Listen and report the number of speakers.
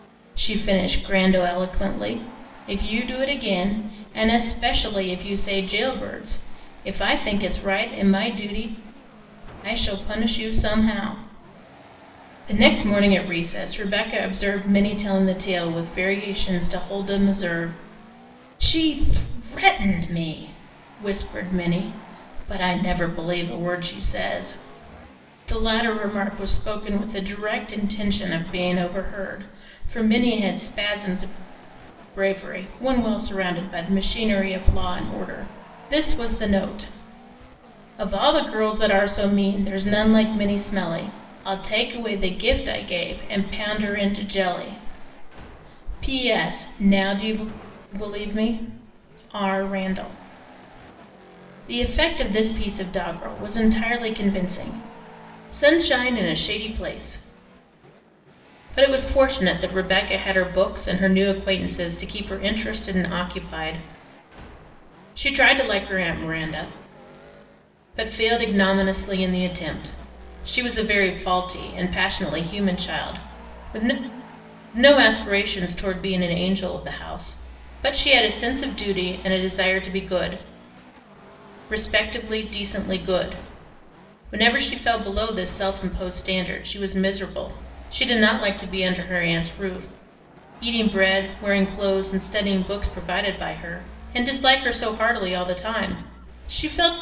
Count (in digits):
1